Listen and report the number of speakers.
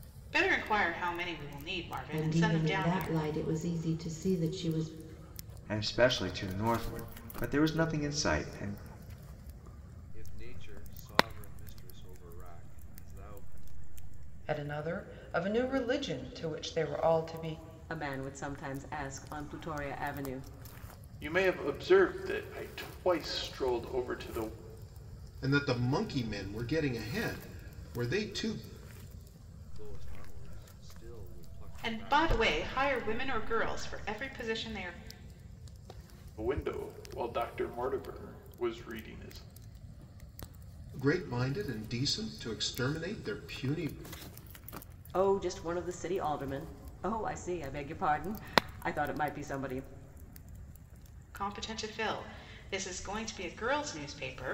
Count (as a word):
eight